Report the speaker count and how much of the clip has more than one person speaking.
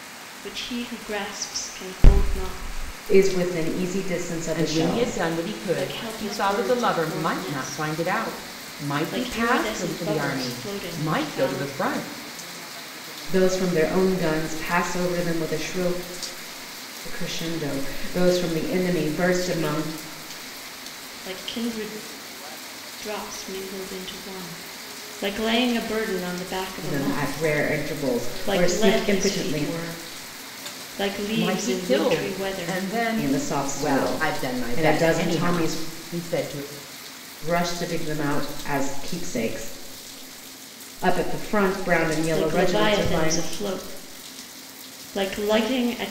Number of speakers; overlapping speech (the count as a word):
three, about 29%